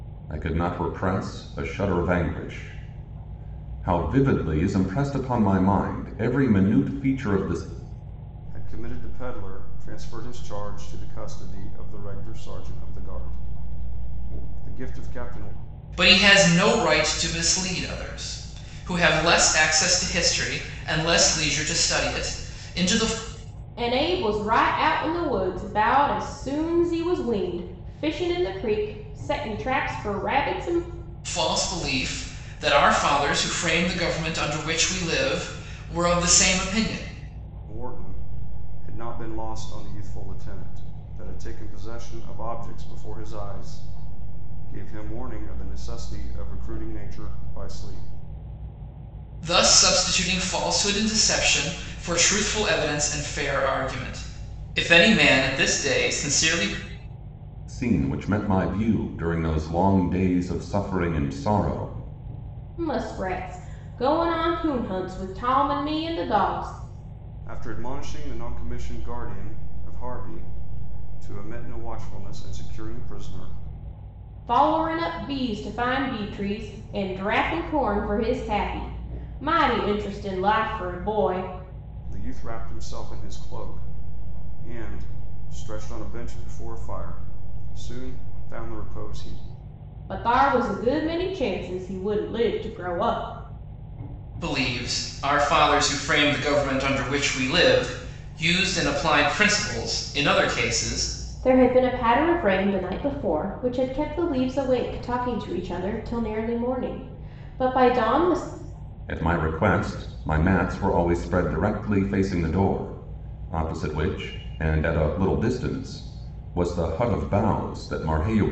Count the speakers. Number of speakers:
4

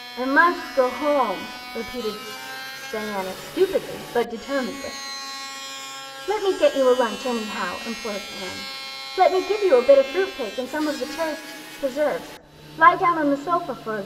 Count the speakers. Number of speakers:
1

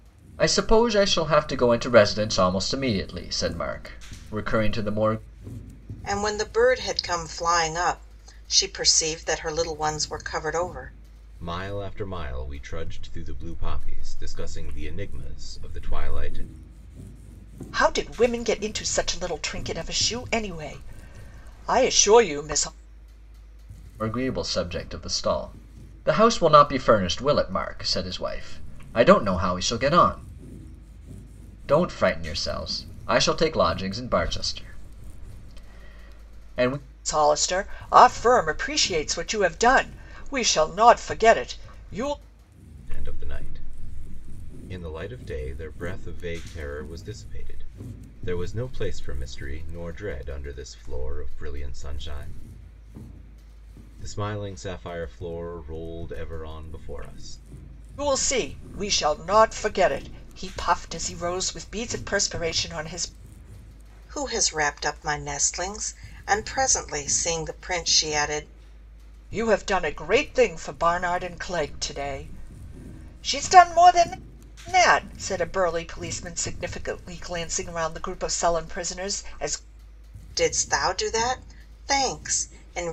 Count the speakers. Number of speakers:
4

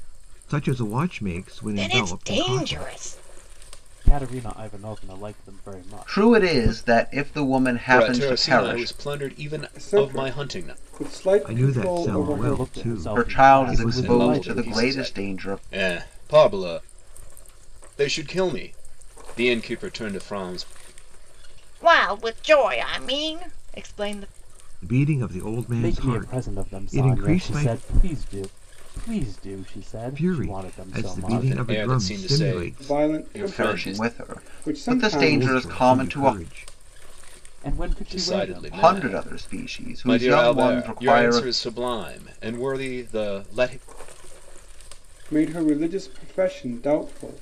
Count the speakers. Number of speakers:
6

